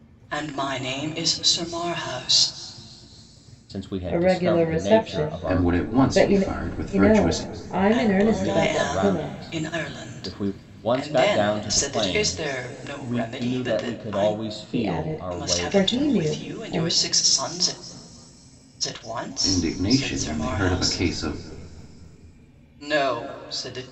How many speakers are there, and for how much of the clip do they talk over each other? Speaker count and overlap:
4, about 54%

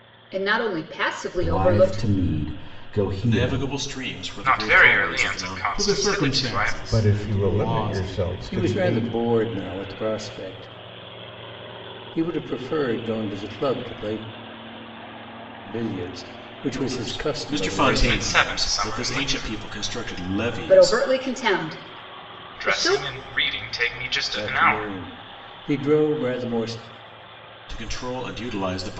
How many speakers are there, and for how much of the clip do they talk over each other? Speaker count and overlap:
7, about 34%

